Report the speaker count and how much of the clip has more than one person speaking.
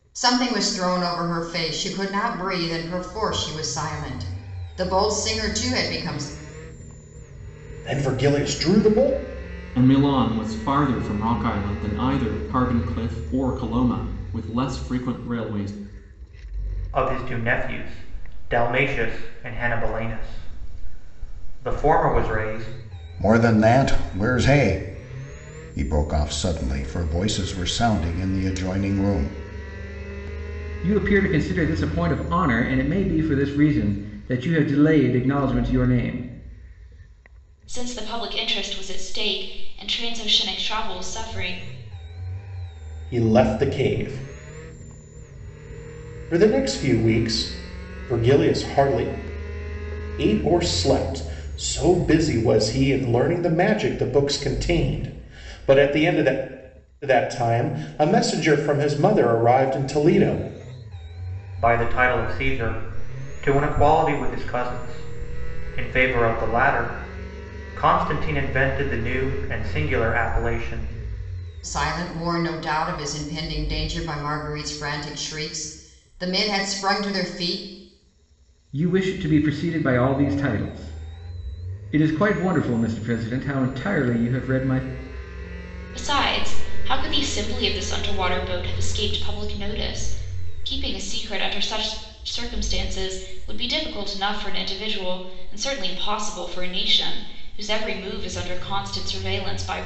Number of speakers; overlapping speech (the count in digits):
7, no overlap